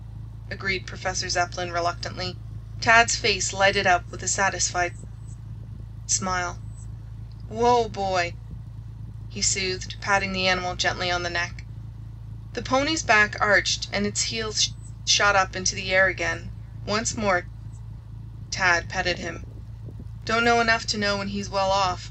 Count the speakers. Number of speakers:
one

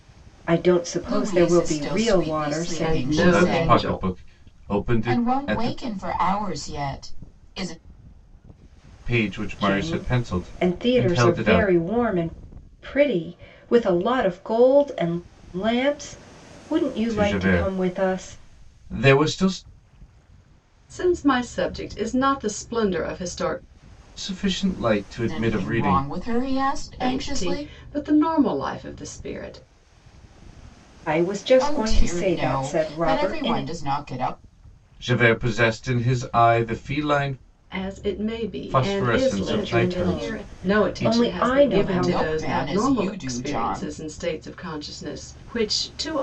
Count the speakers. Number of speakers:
four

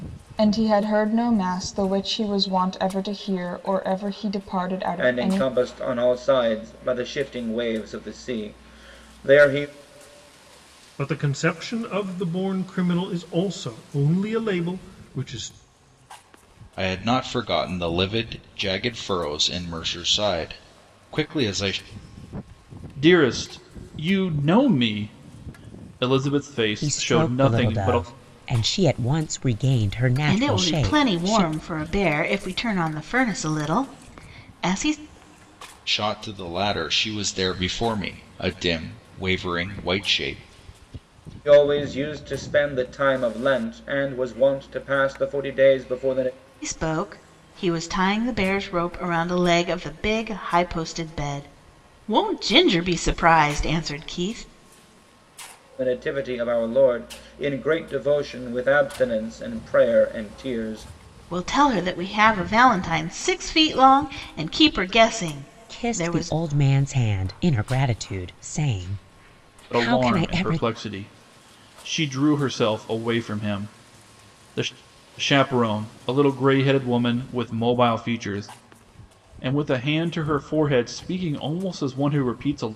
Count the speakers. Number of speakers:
seven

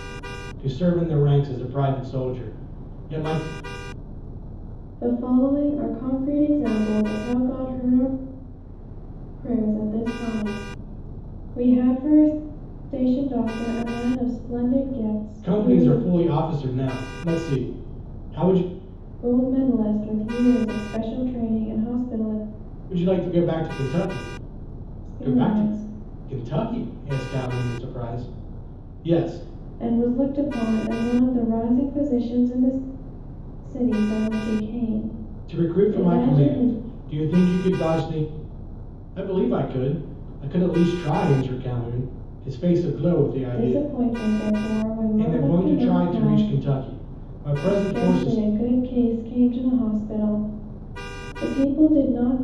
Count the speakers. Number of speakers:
two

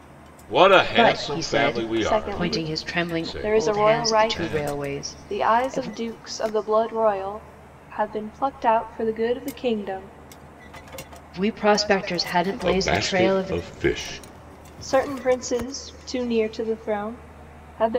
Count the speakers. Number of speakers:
three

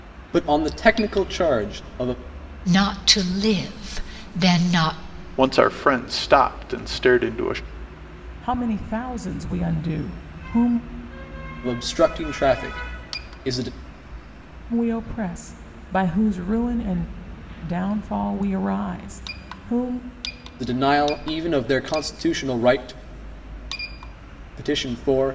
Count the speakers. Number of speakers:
four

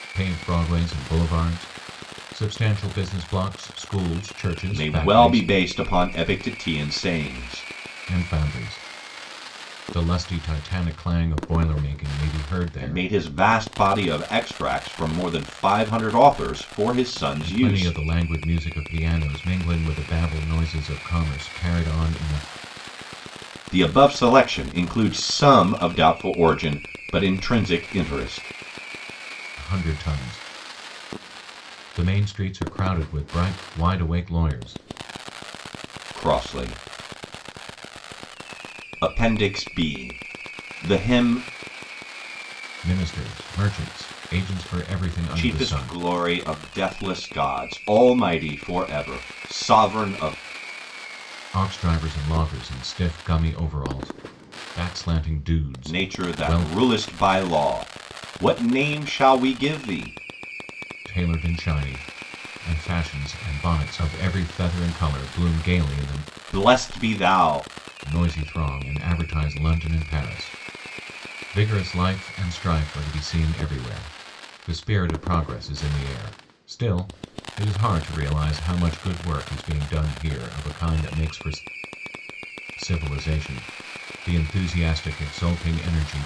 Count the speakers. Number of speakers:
two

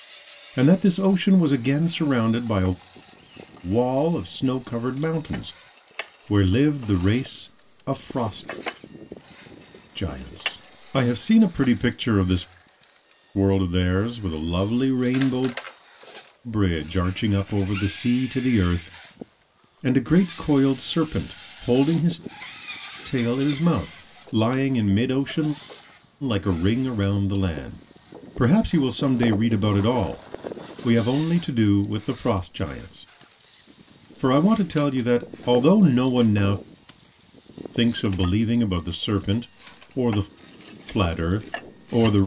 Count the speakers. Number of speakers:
one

